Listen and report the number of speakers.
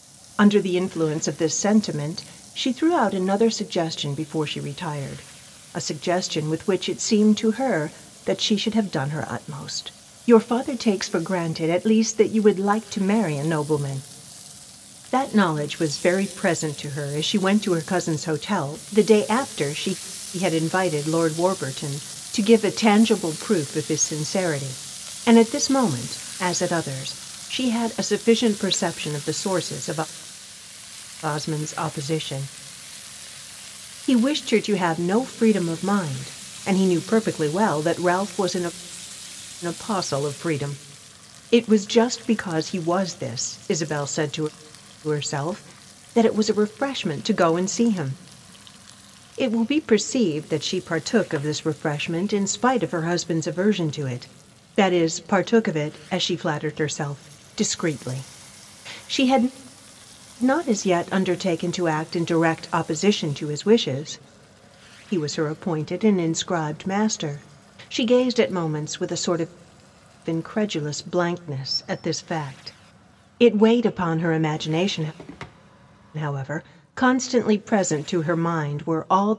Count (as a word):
one